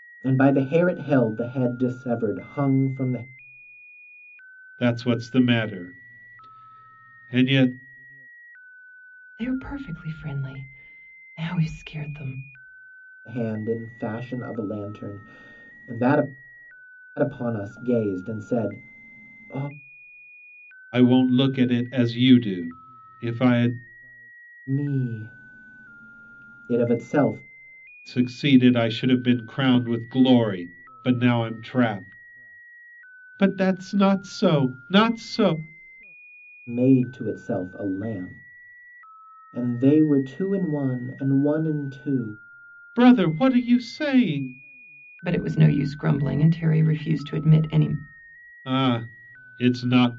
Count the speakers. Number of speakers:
3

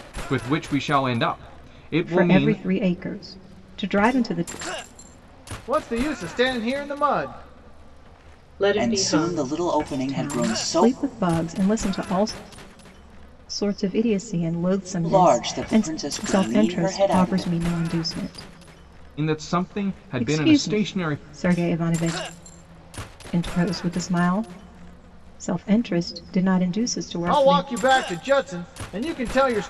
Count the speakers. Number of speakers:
5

